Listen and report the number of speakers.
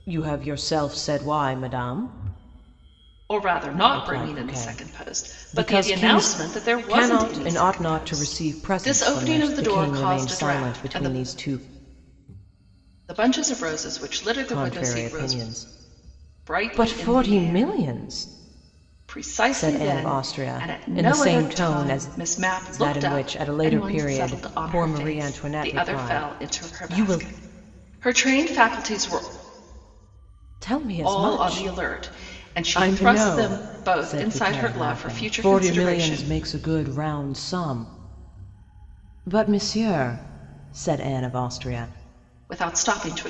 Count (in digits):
2